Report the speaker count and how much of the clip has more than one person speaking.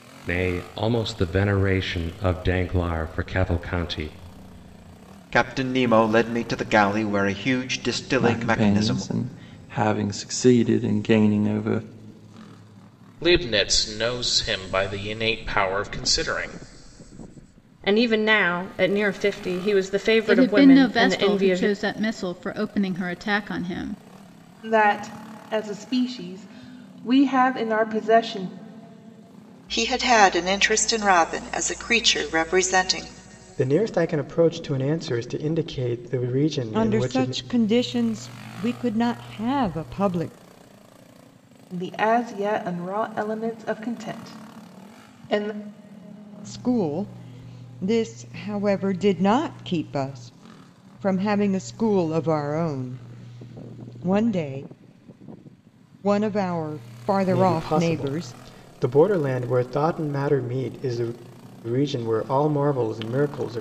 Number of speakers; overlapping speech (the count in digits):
10, about 7%